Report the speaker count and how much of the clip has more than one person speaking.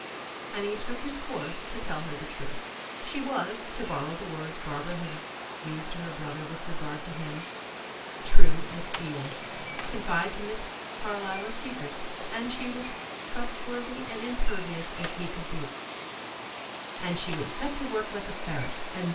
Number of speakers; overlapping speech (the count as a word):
one, no overlap